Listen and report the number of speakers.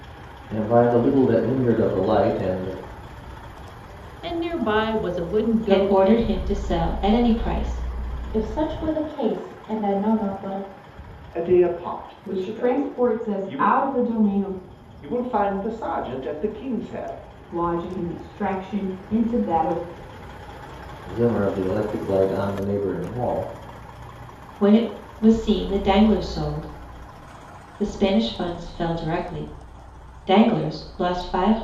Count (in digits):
6